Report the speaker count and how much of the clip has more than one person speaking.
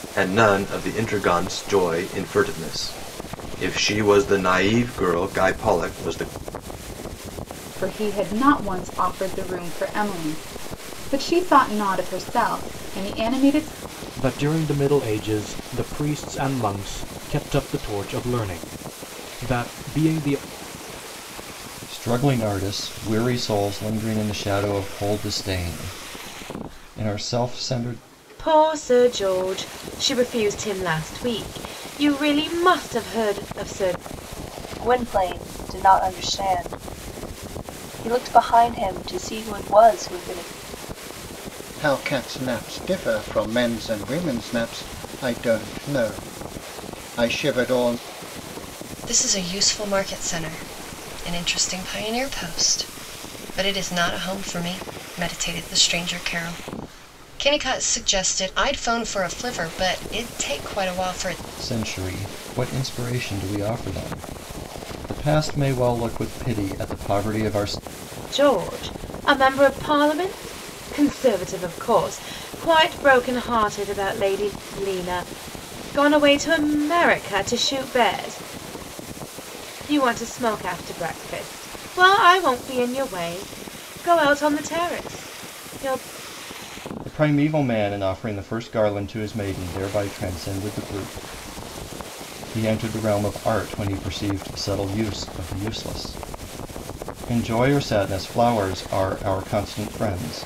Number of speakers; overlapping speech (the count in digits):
8, no overlap